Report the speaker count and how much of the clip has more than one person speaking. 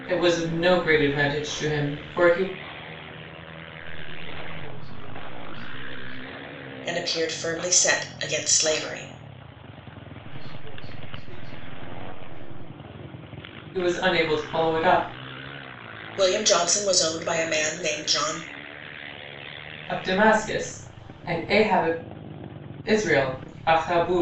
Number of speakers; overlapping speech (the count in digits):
3, no overlap